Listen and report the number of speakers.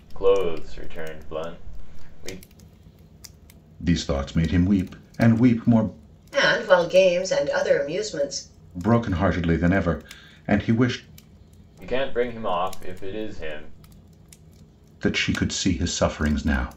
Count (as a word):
three